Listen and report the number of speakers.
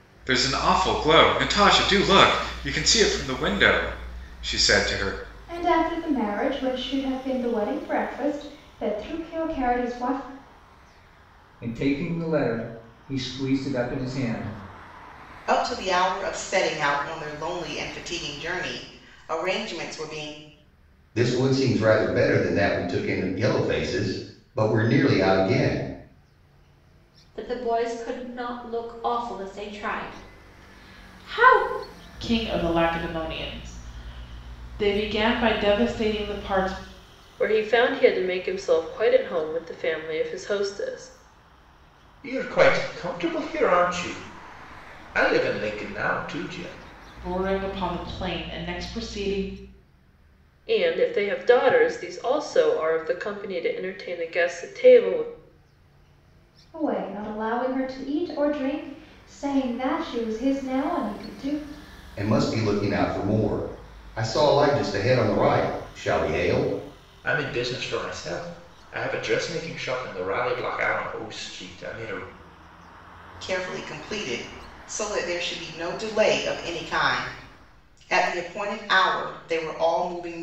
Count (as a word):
nine